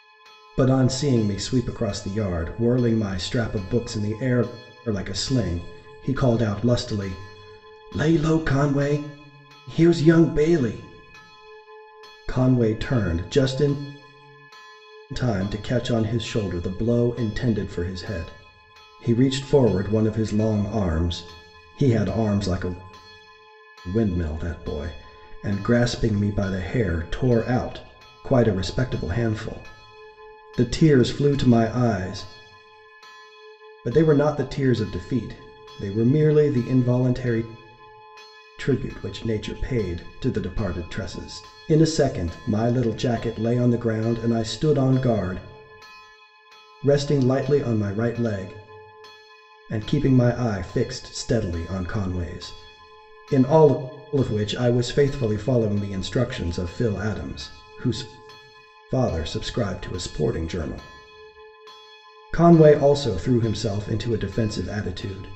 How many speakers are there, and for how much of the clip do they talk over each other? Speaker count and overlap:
1, no overlap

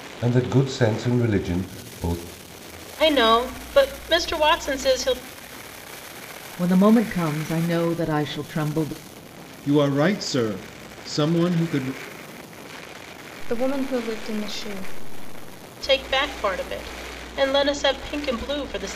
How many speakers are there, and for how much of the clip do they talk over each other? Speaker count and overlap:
5, no overlap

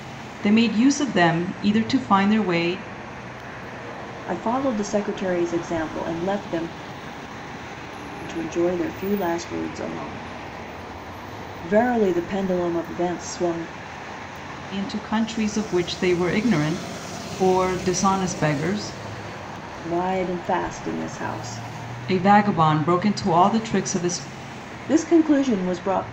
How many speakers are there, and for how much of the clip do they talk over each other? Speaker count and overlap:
2, no overlap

